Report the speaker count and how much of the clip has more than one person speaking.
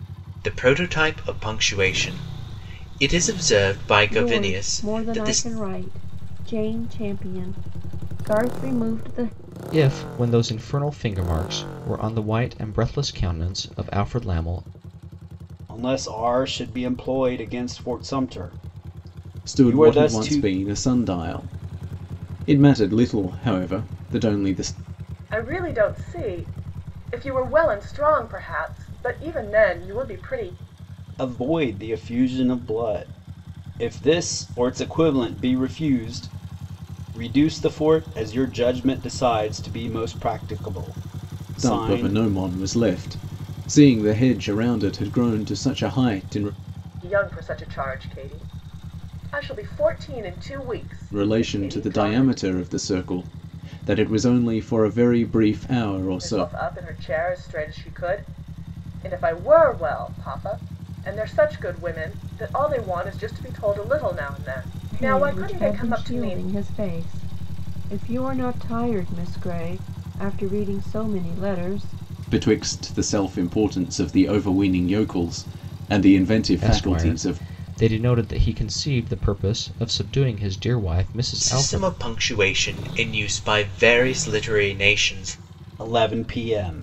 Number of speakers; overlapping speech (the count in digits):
6, about 8%